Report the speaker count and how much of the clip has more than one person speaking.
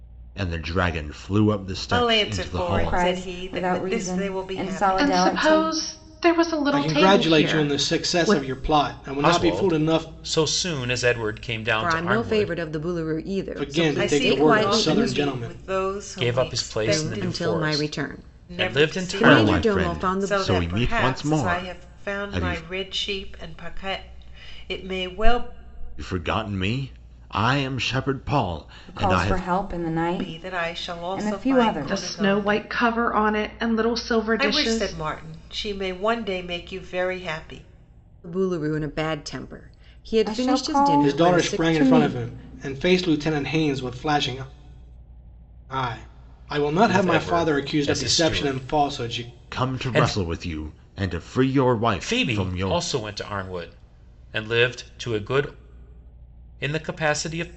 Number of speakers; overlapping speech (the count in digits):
7, about 45%